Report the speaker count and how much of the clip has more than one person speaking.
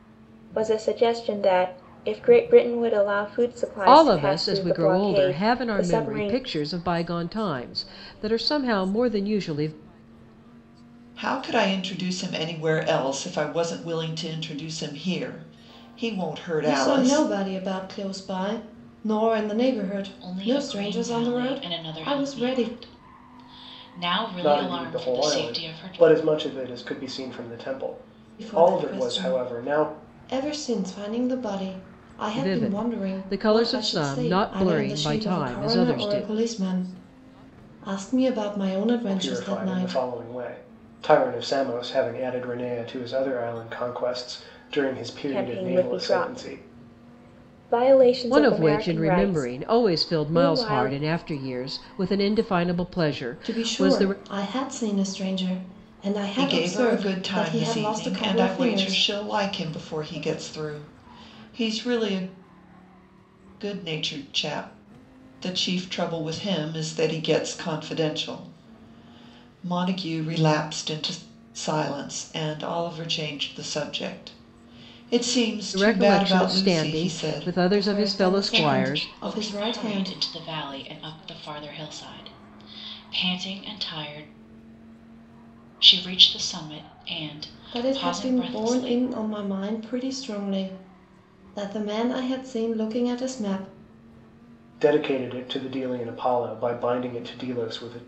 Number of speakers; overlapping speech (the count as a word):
six, about 27%